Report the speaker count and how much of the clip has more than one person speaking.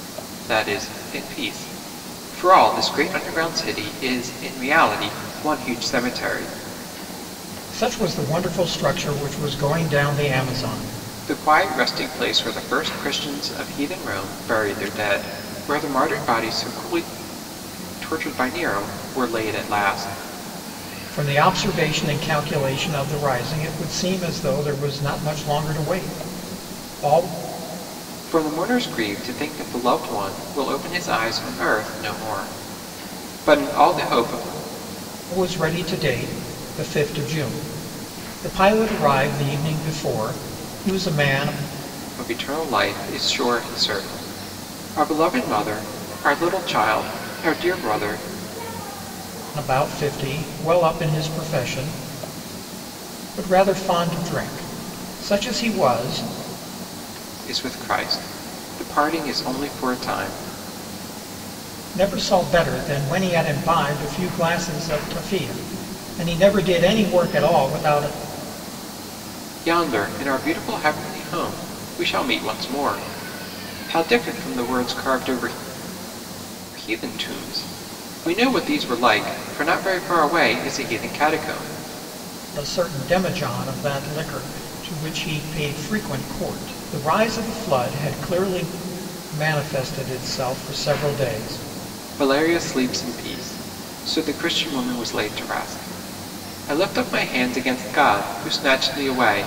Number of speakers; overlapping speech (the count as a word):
two, no overlap